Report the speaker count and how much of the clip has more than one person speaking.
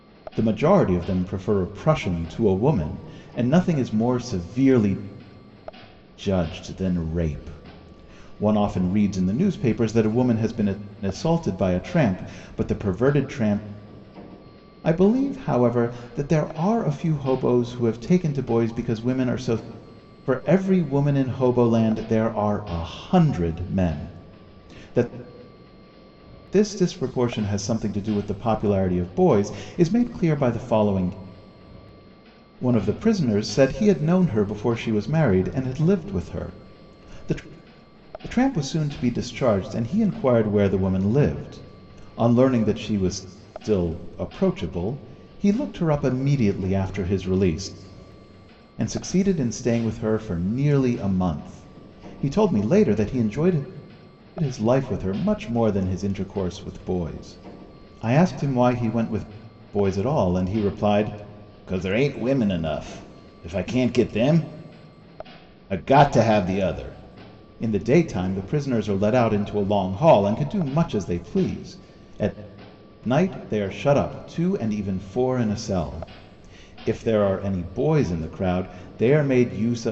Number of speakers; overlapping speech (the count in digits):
1, no overlap